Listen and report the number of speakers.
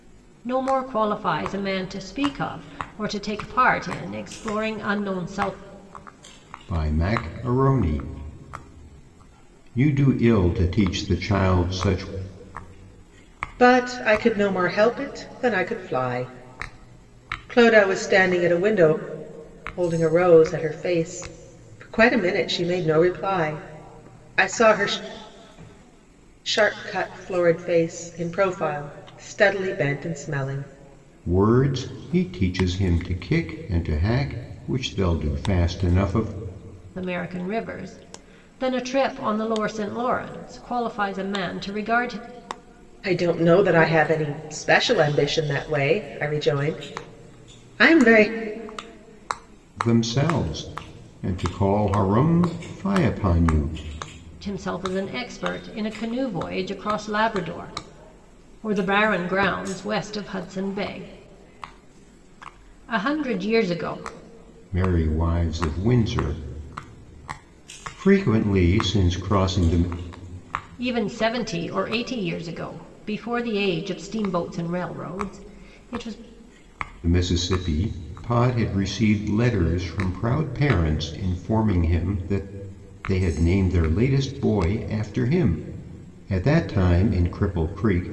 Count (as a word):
three